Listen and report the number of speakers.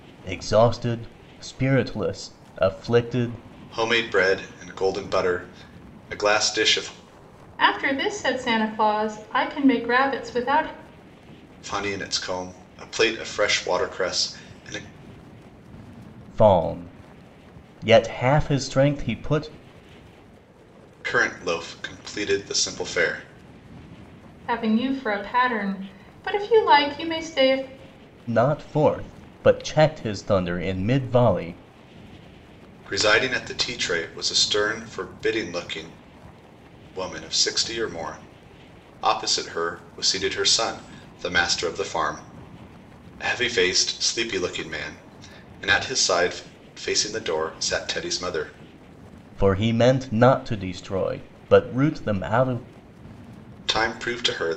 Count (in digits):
3